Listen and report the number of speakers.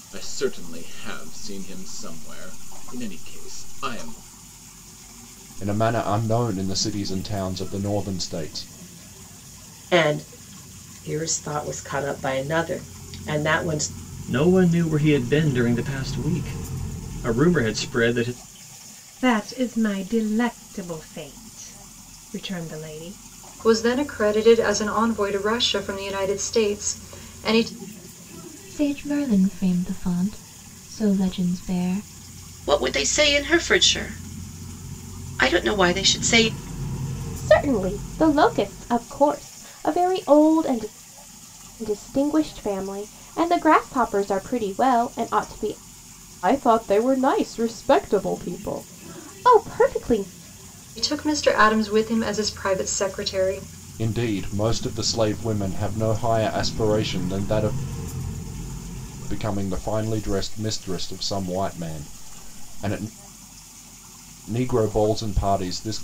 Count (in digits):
9